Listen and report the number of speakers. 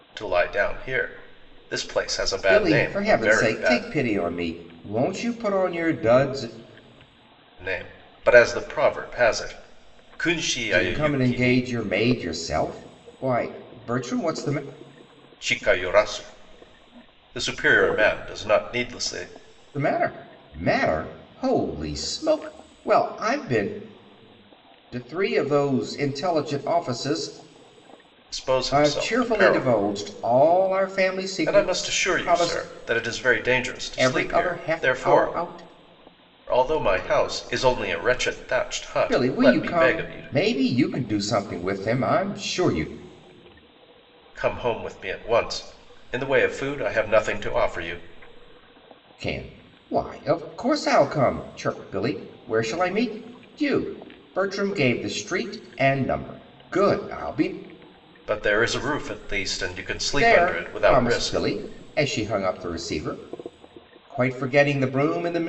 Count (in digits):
2